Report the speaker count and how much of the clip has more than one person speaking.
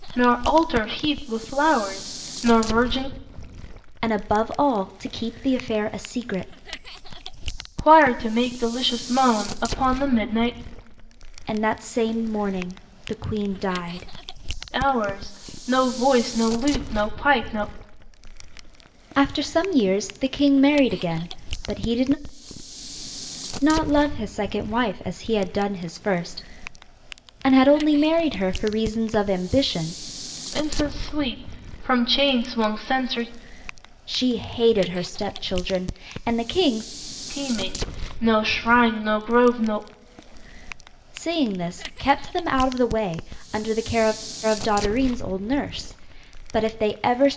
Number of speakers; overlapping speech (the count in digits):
2, no overlap